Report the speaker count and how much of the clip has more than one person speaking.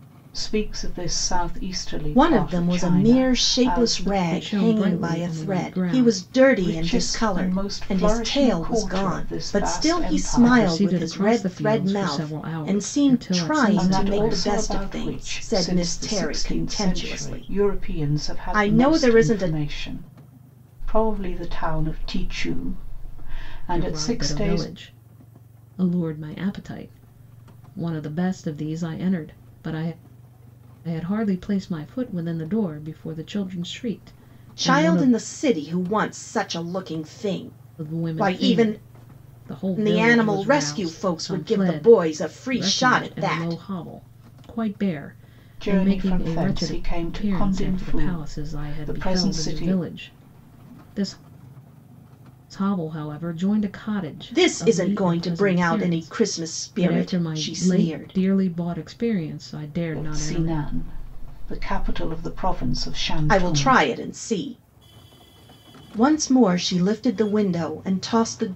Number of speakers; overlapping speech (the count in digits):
3, about 46%